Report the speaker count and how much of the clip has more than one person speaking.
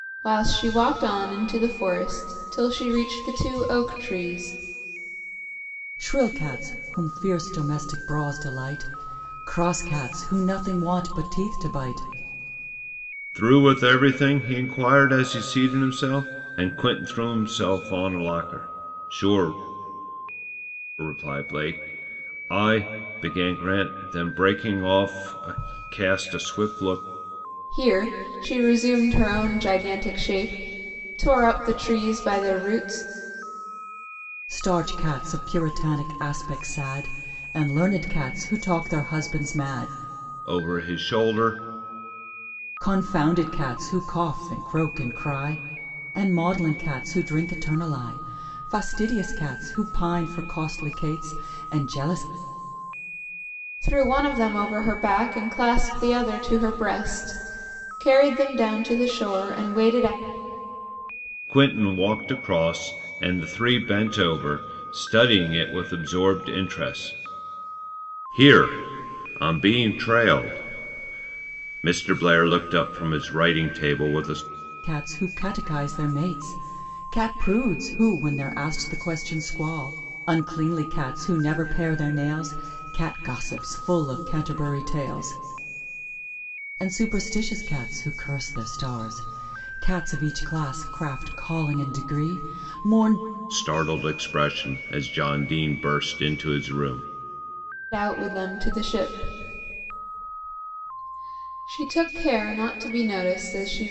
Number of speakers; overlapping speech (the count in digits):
3, no overlap